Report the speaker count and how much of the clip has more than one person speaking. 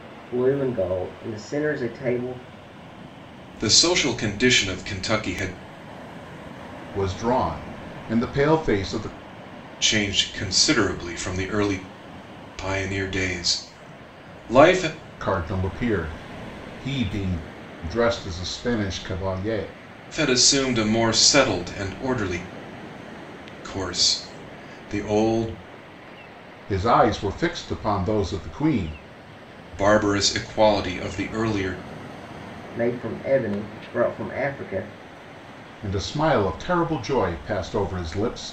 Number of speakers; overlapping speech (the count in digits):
3, no overlap